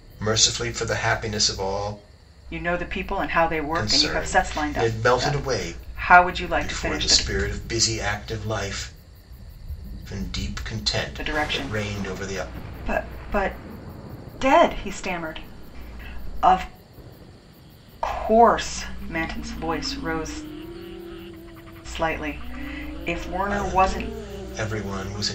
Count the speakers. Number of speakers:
two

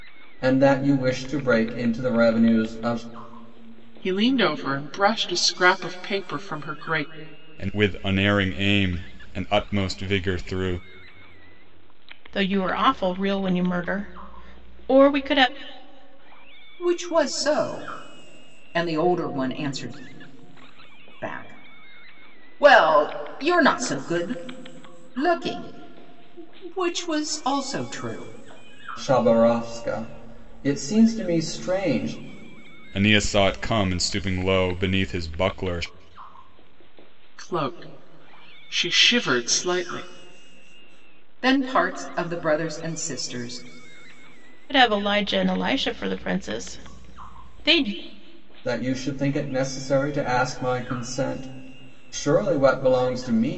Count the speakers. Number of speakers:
five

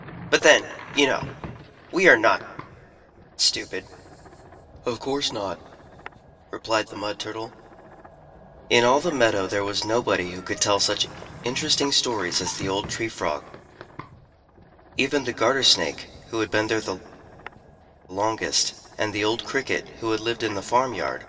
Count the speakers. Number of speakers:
one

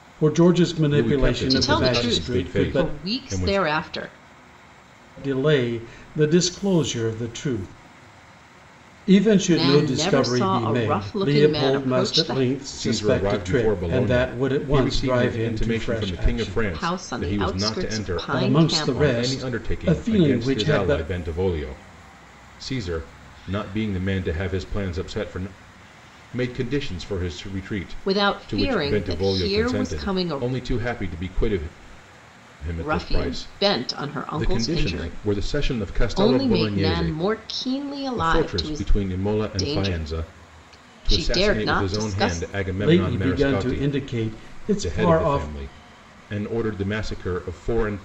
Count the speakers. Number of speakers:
three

